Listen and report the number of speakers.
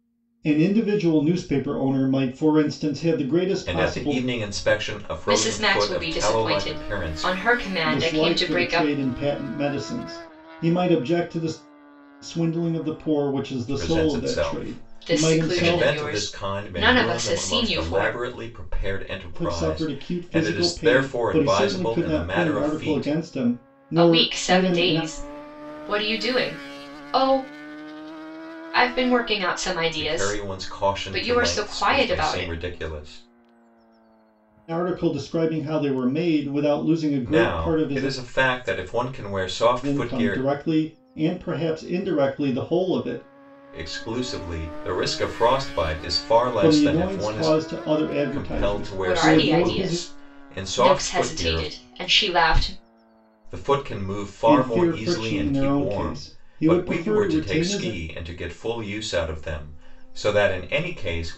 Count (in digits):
3